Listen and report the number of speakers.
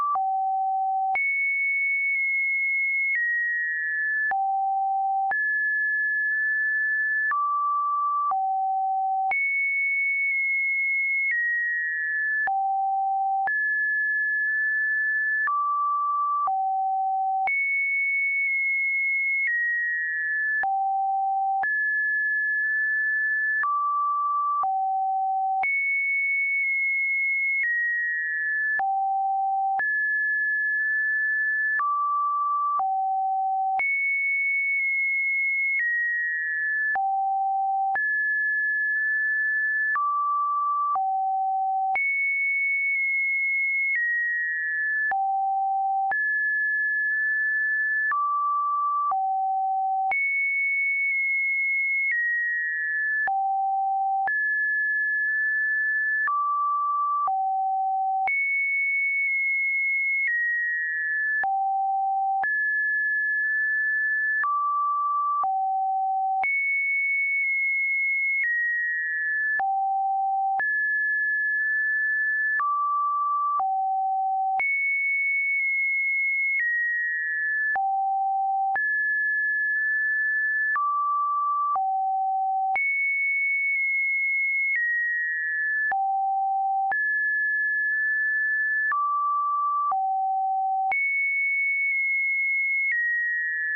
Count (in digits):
0